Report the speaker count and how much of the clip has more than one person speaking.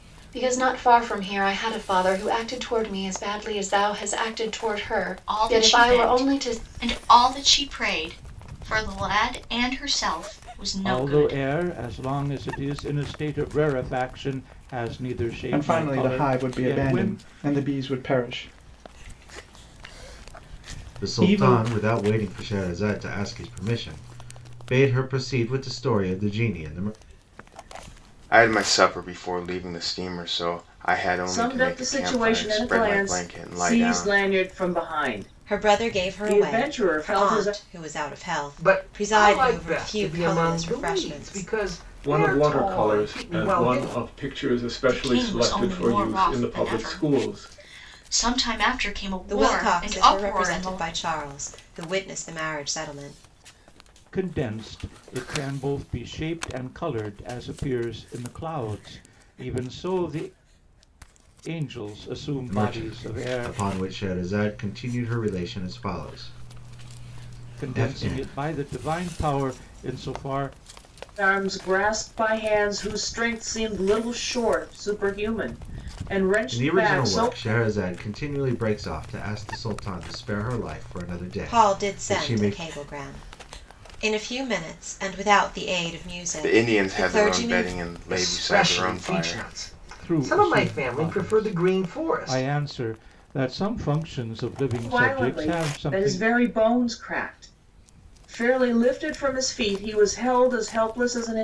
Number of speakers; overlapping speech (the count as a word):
ten, about 29%